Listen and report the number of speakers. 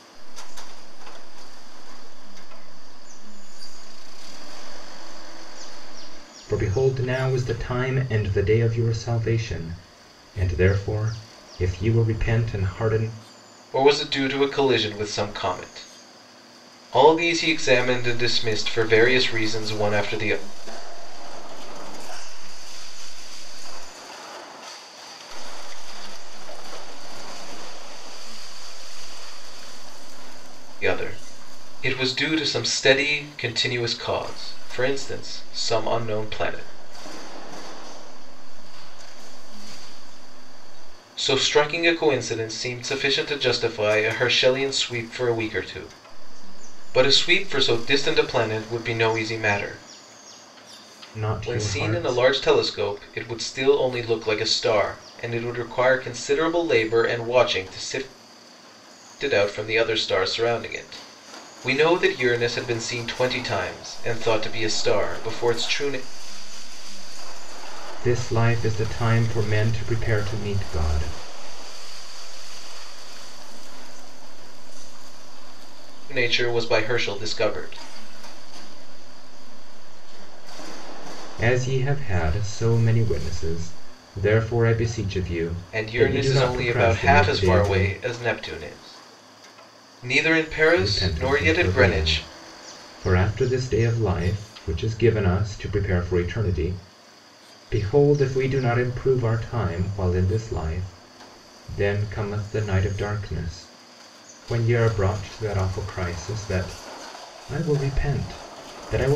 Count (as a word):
three